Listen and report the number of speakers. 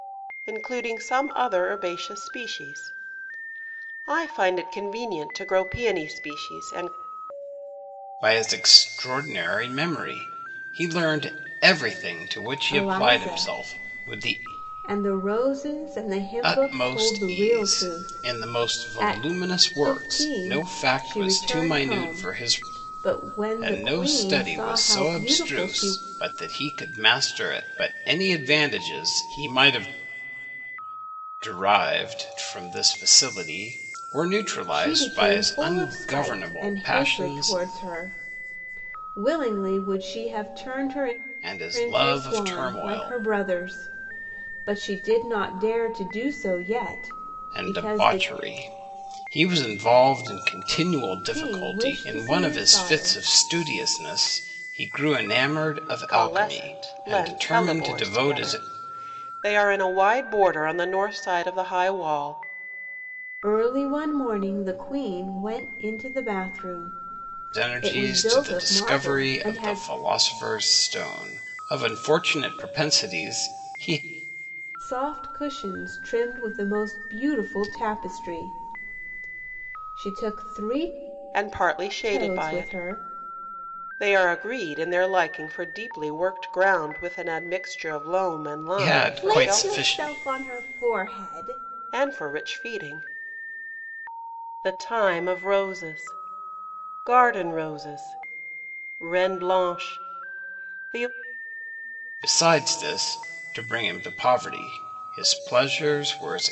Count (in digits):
3